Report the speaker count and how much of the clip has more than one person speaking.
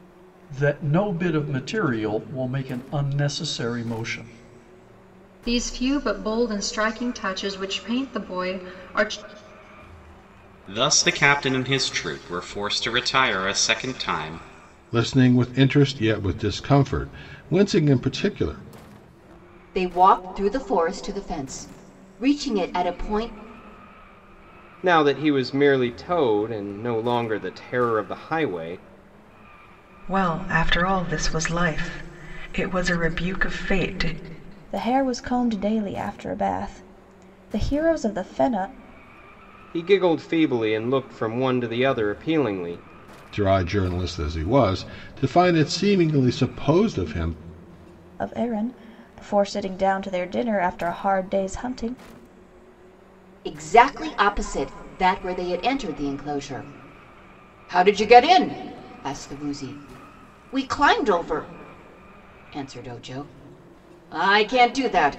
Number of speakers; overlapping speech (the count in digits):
8, no overlap